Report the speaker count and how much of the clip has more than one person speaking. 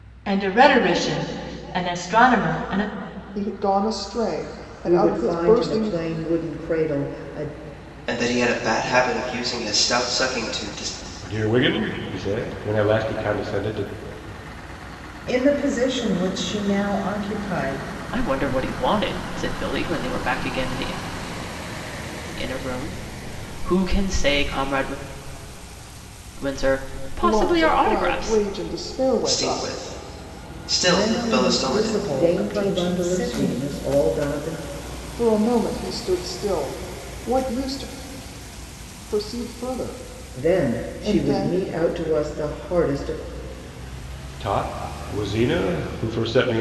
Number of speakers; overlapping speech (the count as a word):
seven, about 14%